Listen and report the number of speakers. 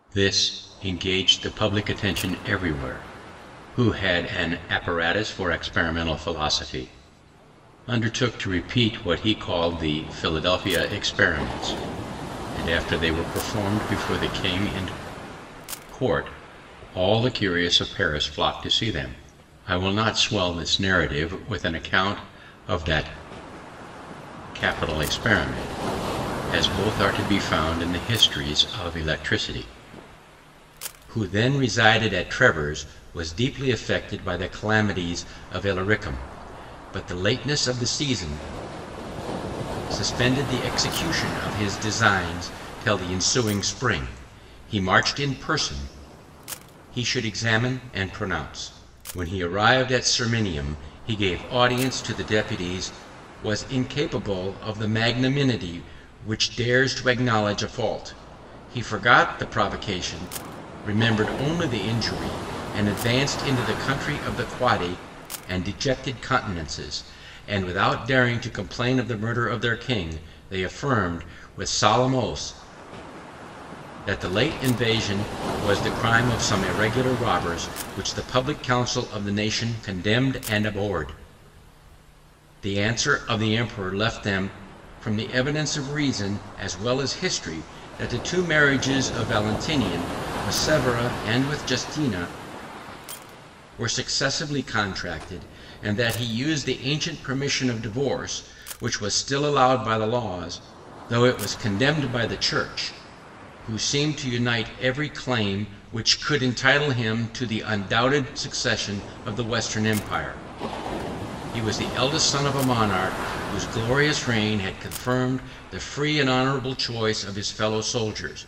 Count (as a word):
one